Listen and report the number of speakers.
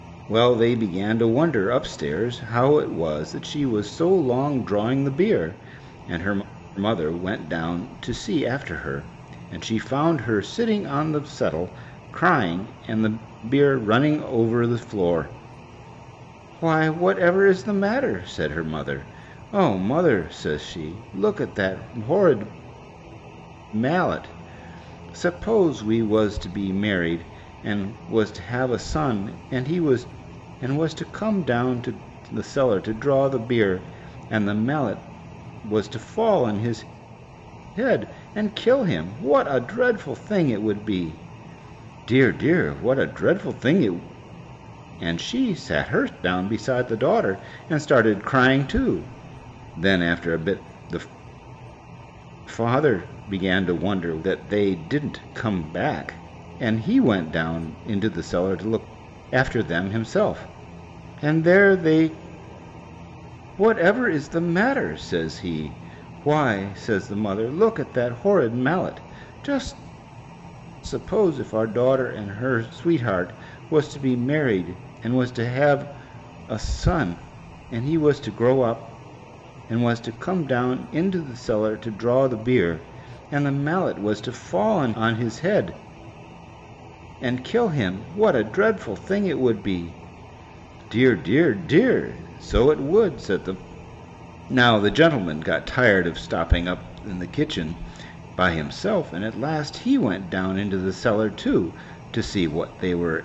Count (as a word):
one